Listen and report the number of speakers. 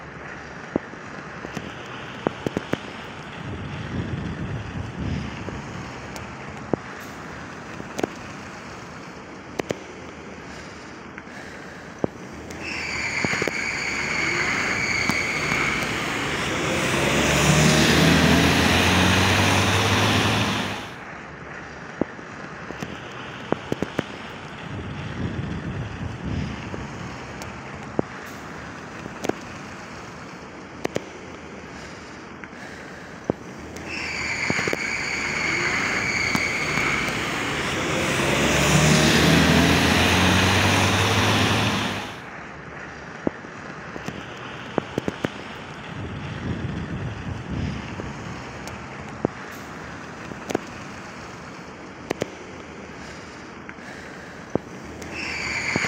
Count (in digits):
0